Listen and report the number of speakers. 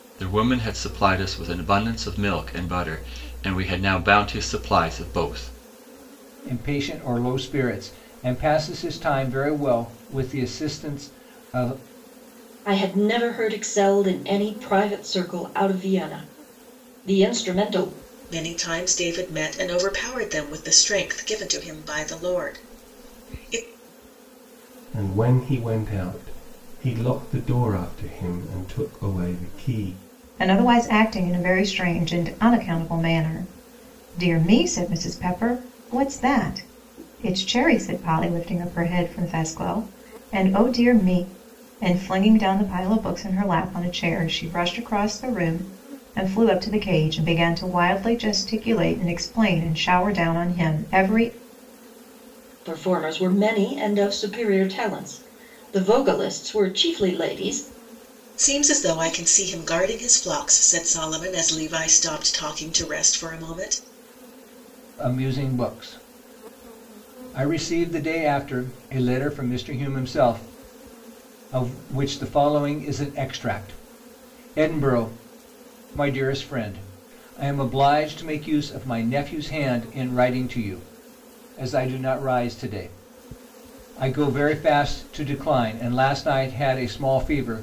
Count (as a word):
six